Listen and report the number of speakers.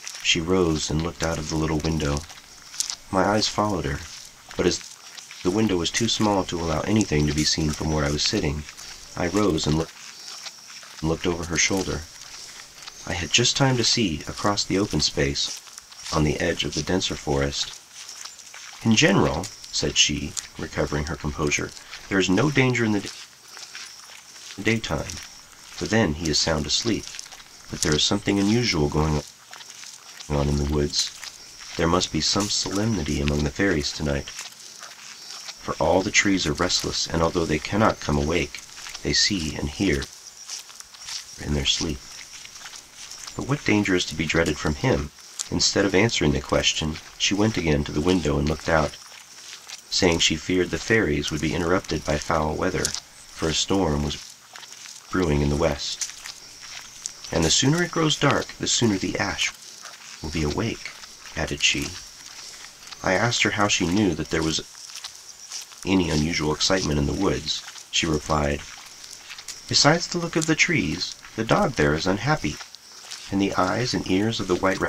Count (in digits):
1